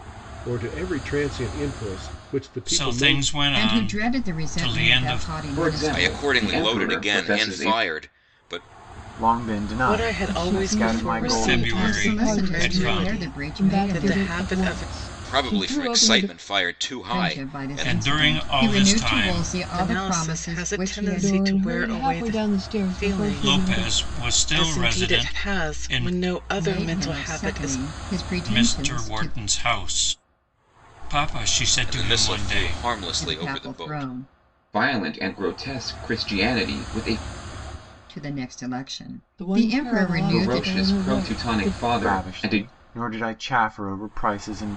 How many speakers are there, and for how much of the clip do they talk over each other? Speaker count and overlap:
eight, about 59%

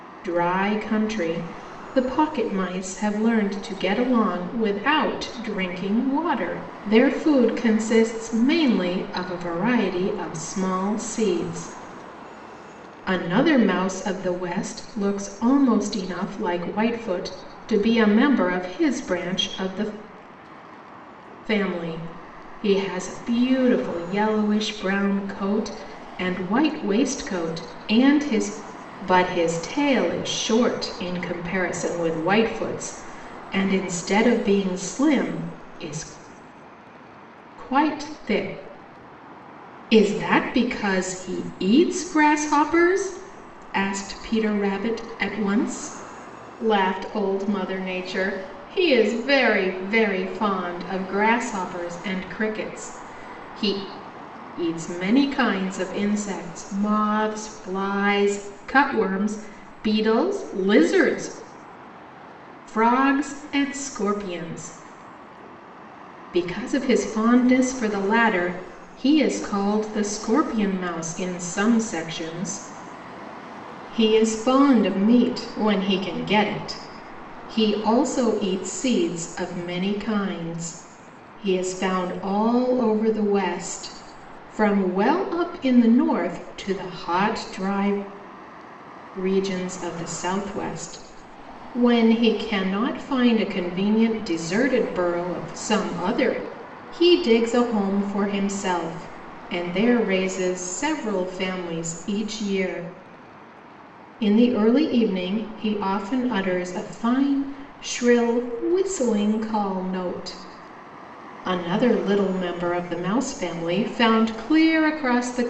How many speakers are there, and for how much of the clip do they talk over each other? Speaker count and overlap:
one, no overlap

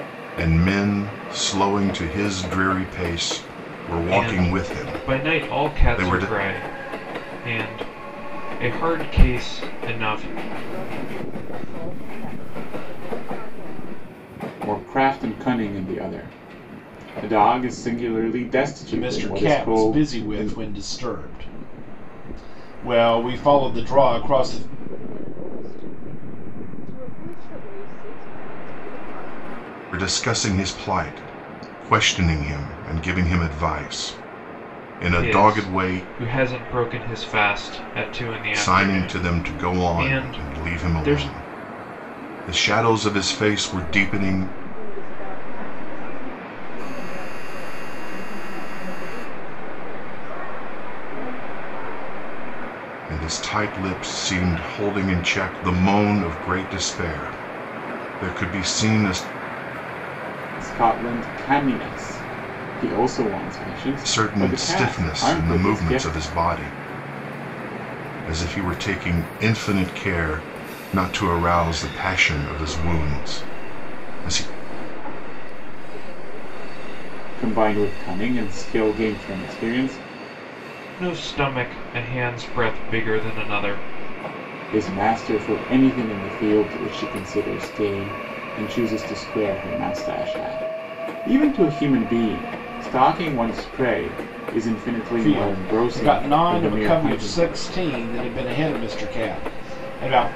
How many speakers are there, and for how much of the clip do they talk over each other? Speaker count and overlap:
five, about 21%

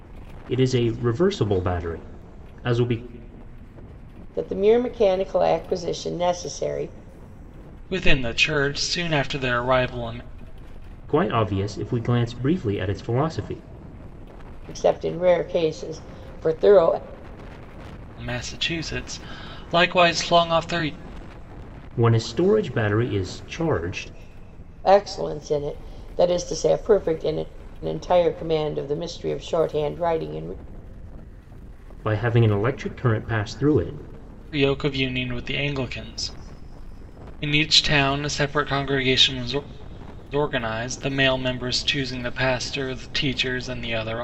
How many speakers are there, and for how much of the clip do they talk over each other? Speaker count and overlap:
three, no overlap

